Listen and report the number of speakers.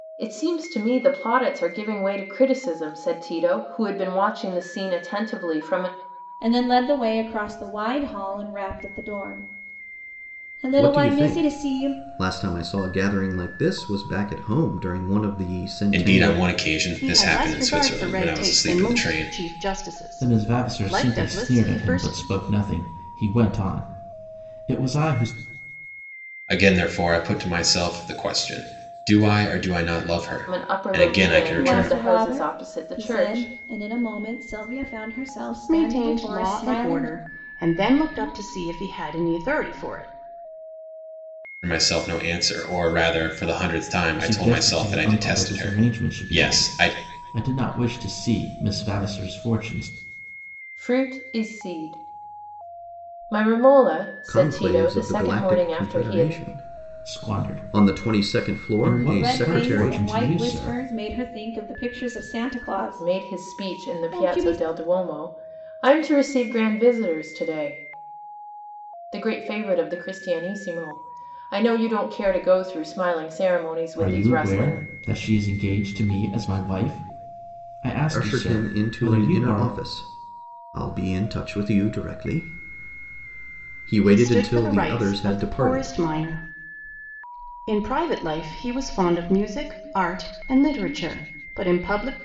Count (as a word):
six